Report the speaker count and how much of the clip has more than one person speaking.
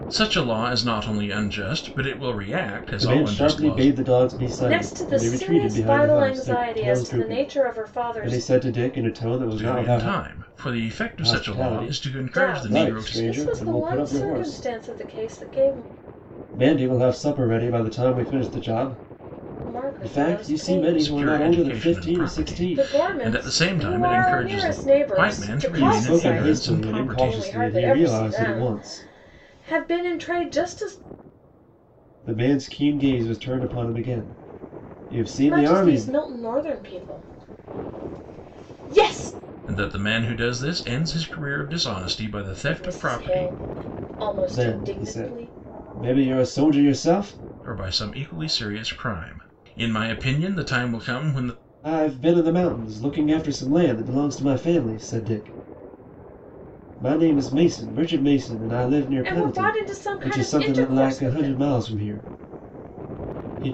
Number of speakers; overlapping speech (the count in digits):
3, about 36%